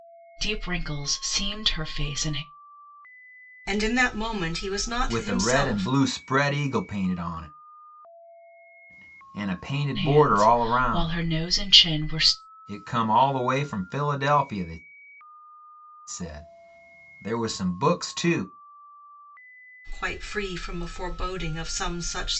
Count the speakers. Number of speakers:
3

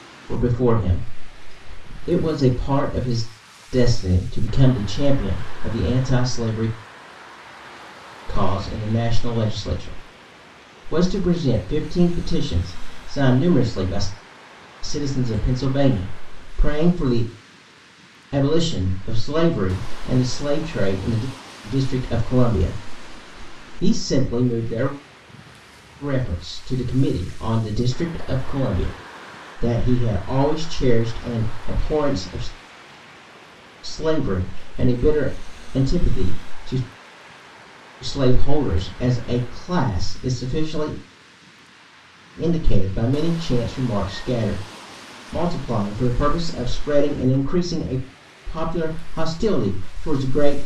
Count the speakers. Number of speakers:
1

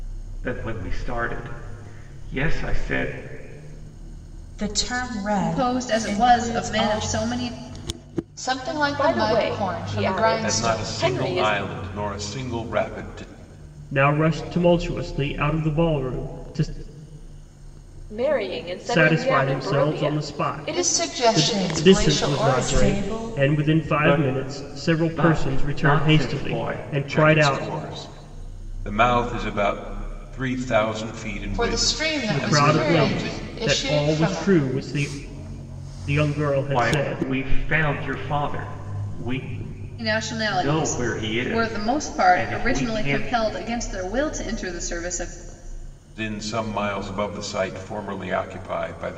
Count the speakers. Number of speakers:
7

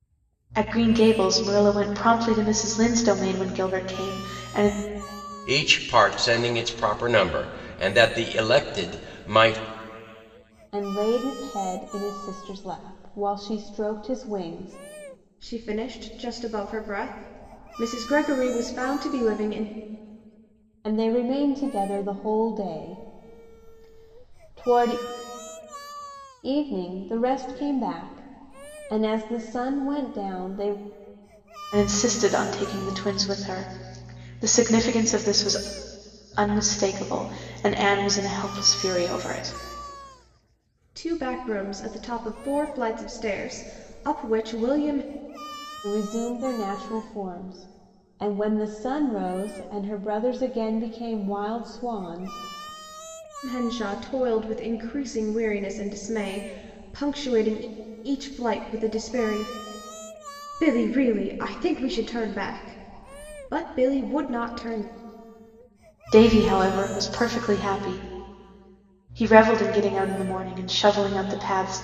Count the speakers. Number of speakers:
4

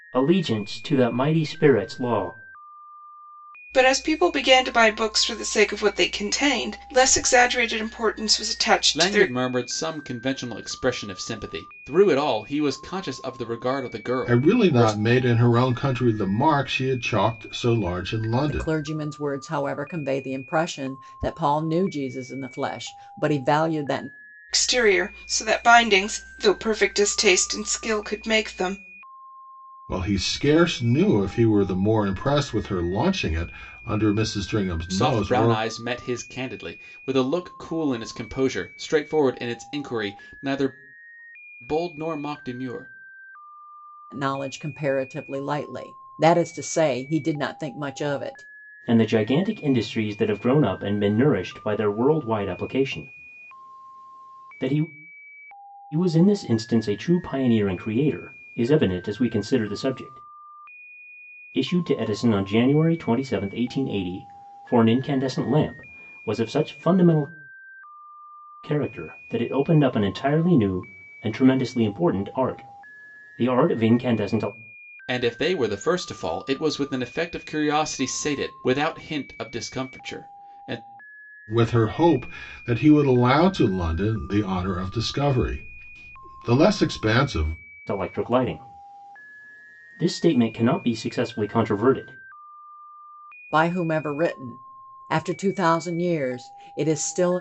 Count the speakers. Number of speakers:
5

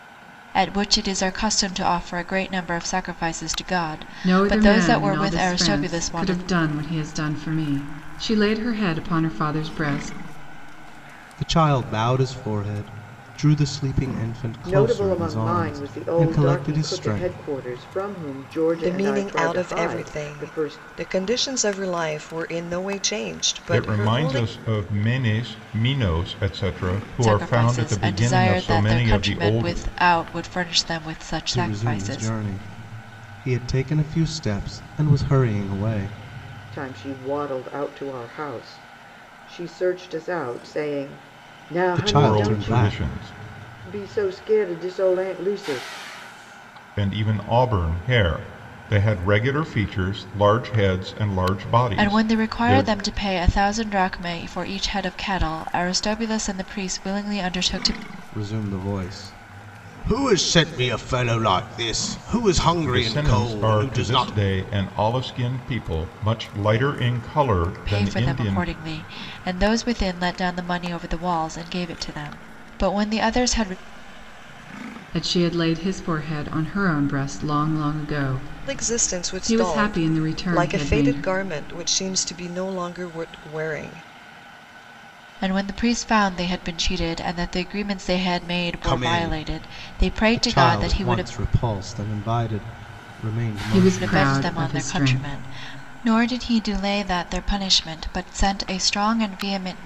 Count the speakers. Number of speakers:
6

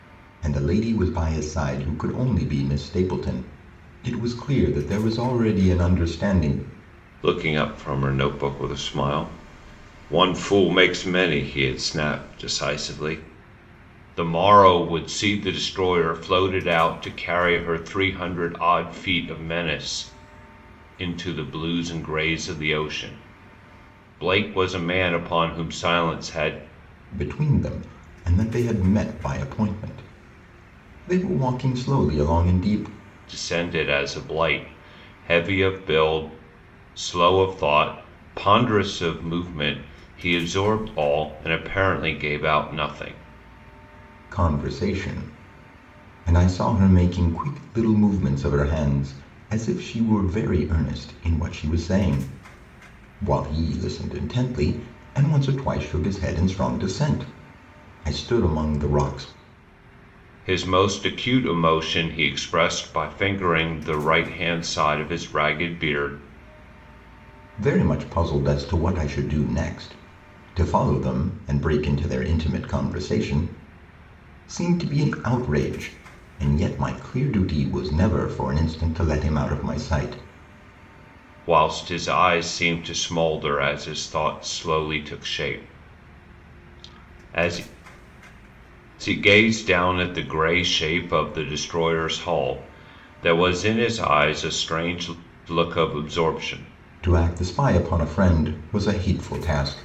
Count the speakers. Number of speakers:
2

